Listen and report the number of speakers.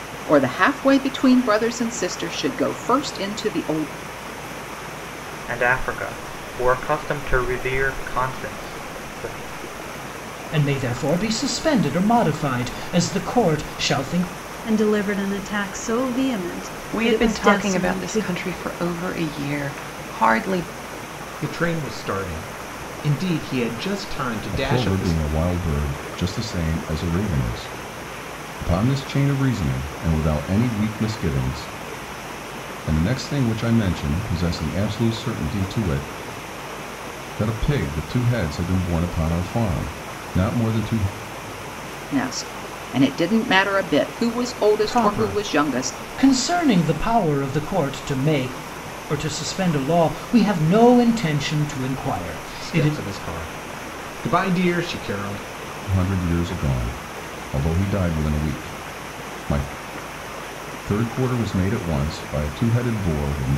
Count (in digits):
7